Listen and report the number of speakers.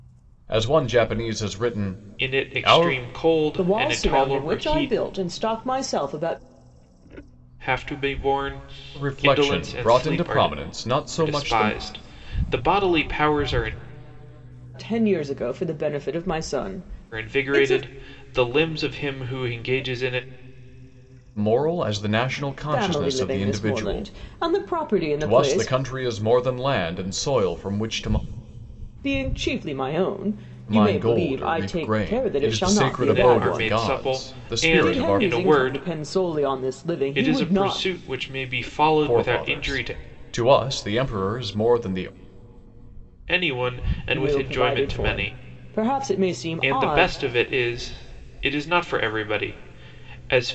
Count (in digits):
3